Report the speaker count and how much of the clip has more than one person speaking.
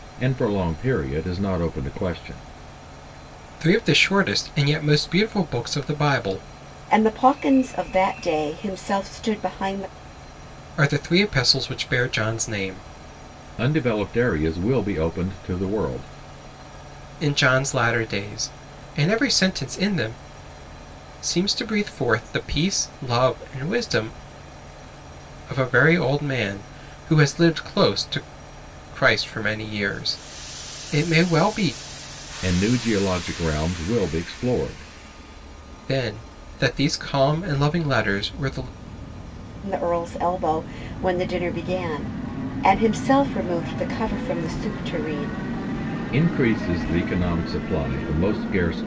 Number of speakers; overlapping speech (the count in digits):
3, no overlap